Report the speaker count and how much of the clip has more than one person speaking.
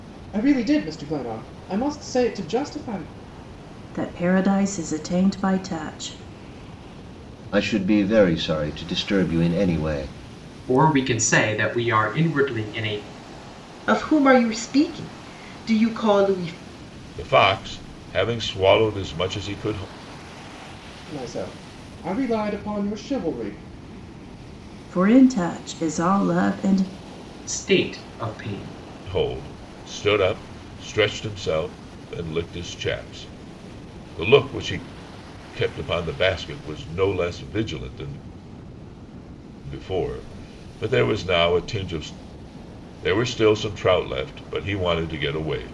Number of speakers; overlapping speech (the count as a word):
six, no overlap